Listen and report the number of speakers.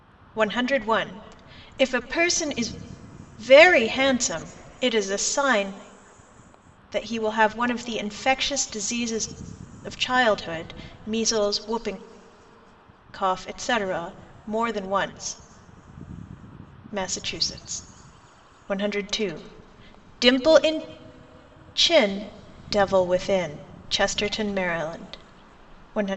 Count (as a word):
one